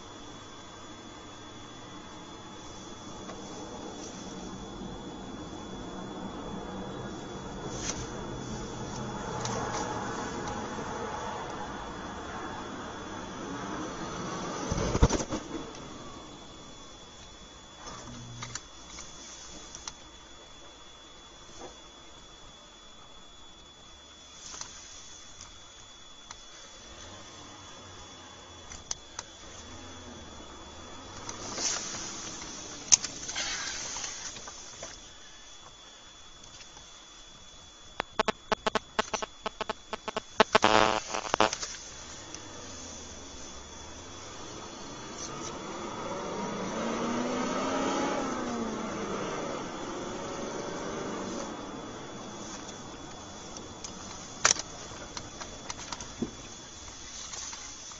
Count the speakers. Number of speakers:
zero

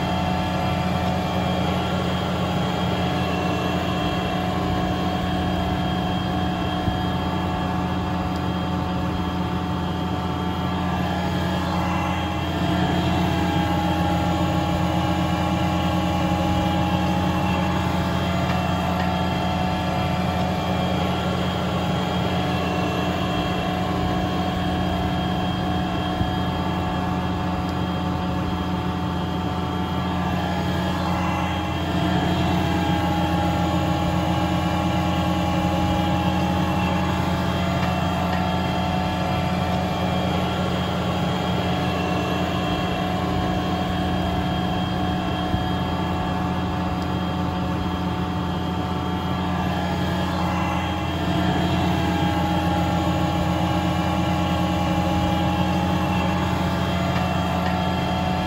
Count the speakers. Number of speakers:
zero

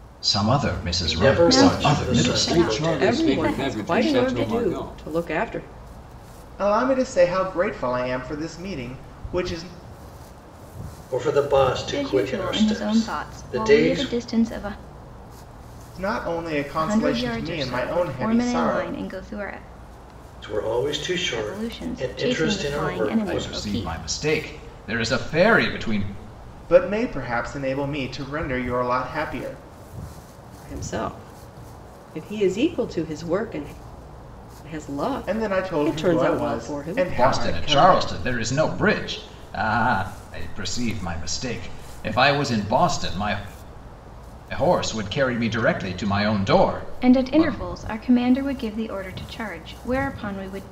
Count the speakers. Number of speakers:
six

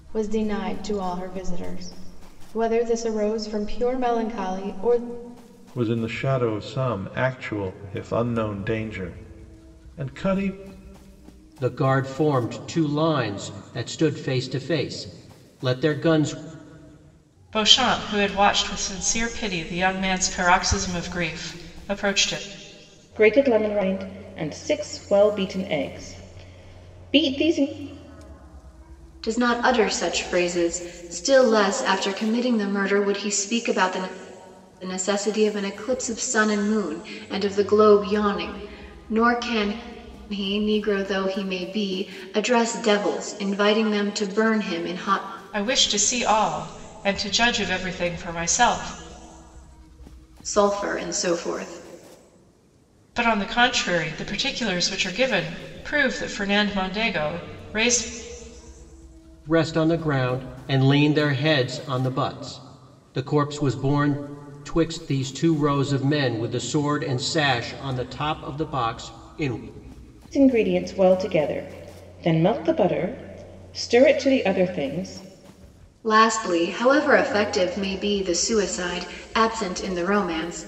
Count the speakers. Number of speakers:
six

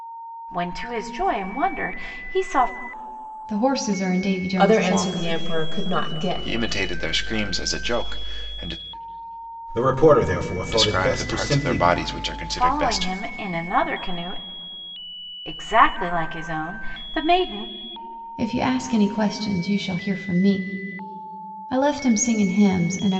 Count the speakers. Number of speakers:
six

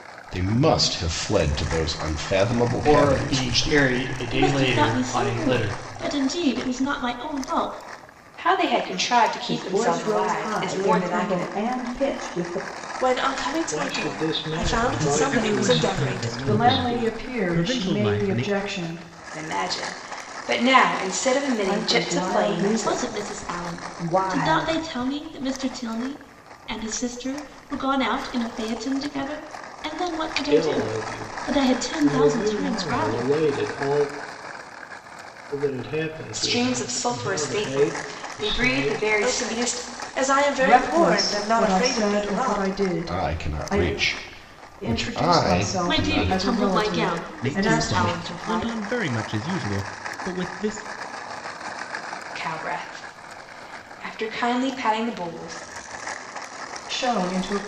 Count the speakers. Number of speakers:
nine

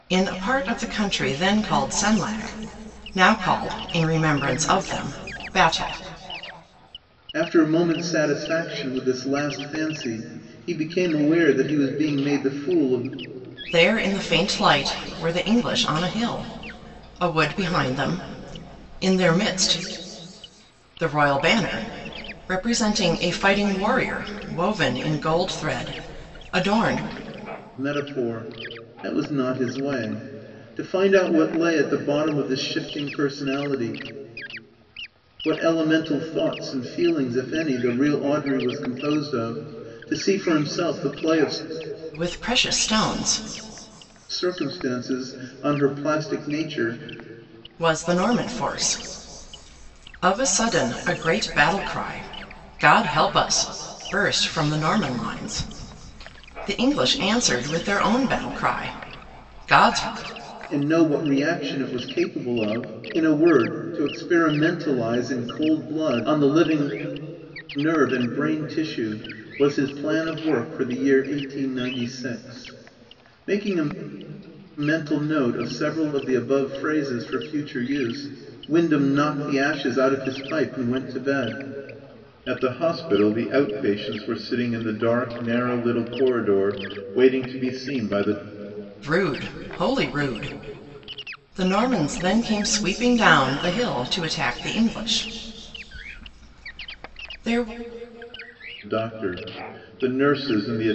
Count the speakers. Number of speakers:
two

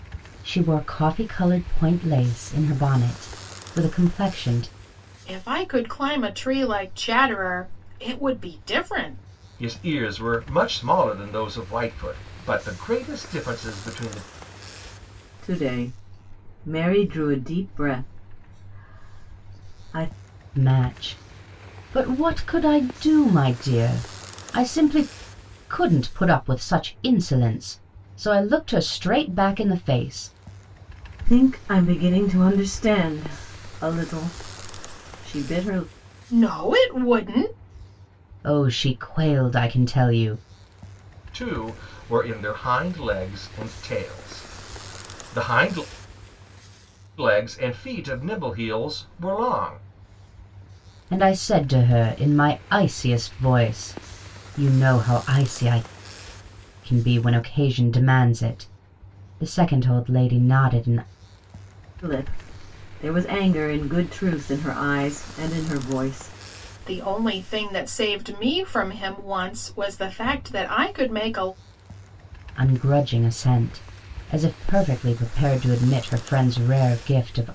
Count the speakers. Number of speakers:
four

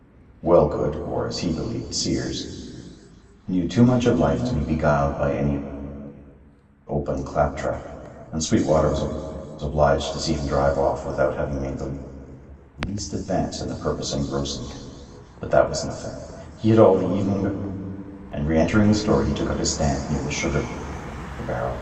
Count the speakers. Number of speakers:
one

